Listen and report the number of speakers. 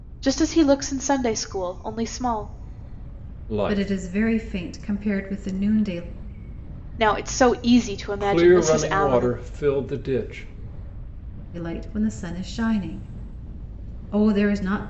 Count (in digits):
3